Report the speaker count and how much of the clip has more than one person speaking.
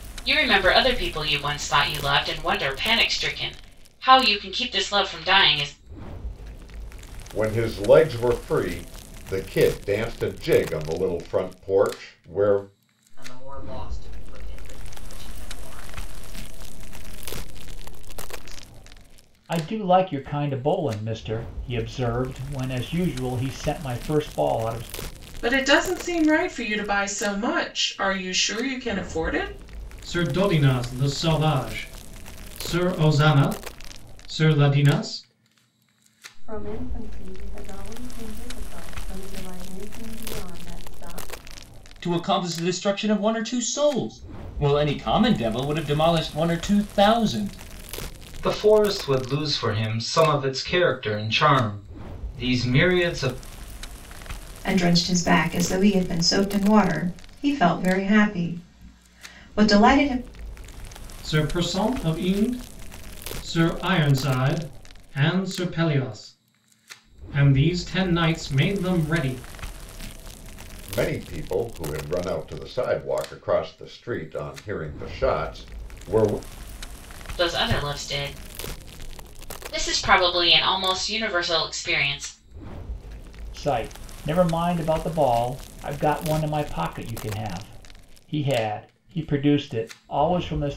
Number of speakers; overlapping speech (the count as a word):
ten, no overlap